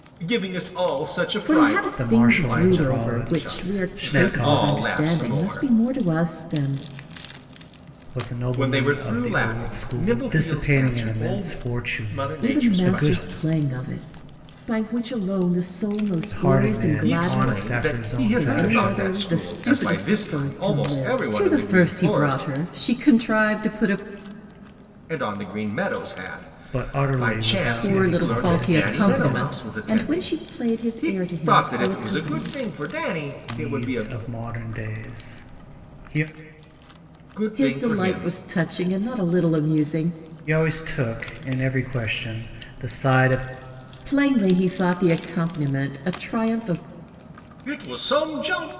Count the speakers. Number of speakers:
3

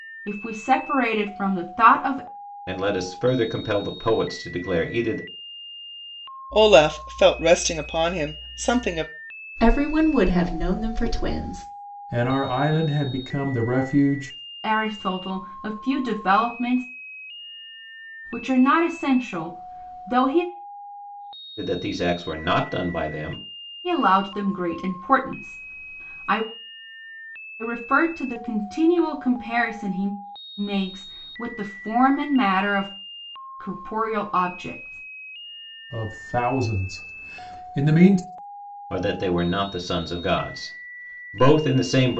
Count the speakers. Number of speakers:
5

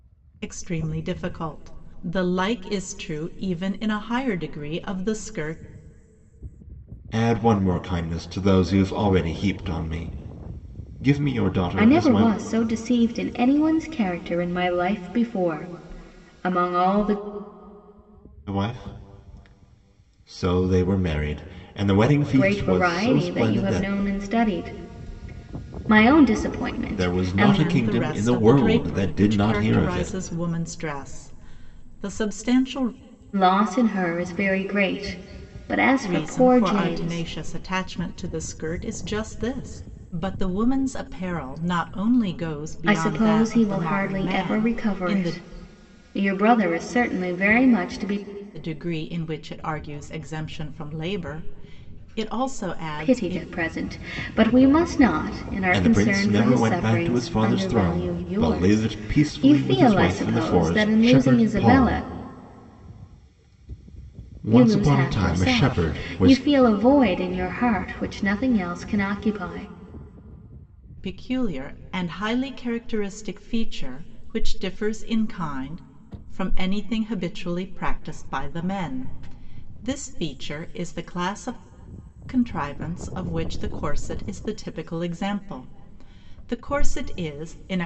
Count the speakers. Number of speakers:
3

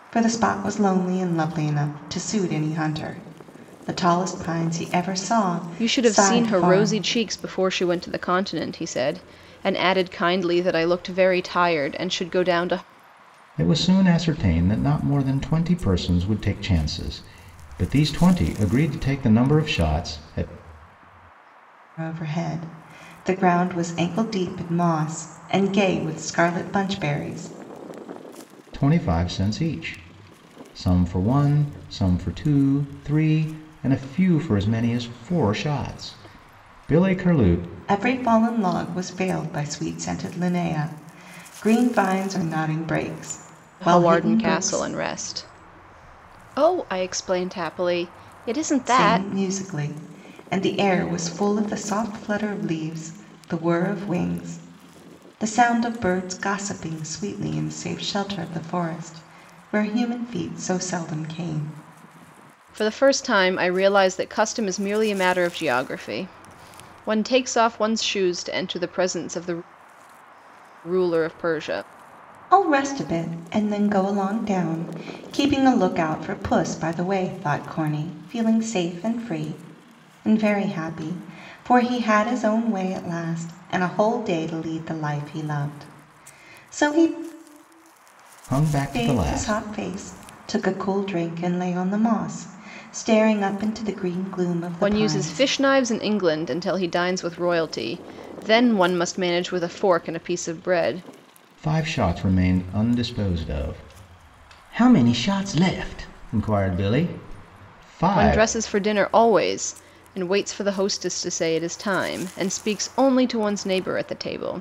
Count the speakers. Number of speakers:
3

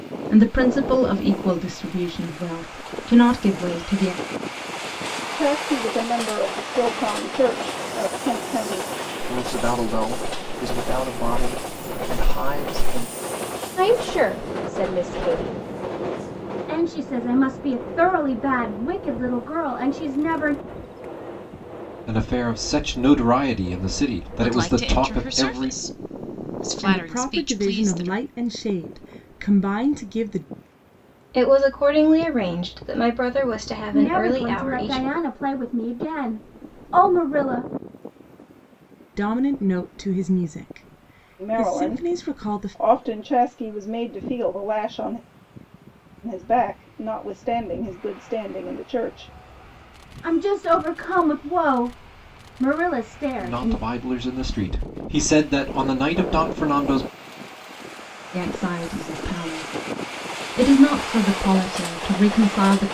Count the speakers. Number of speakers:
9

